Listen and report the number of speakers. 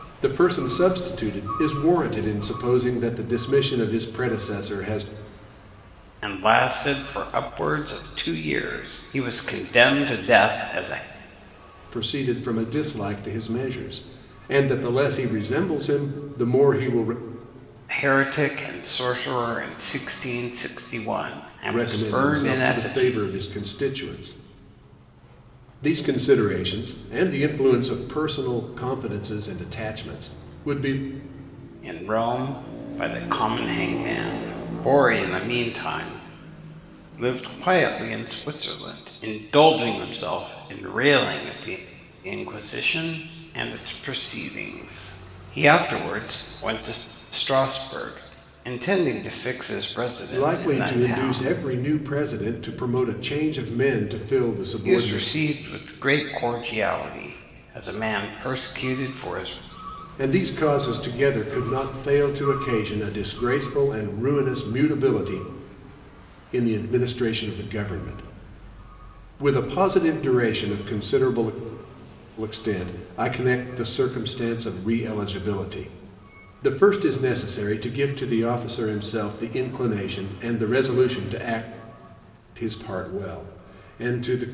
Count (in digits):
2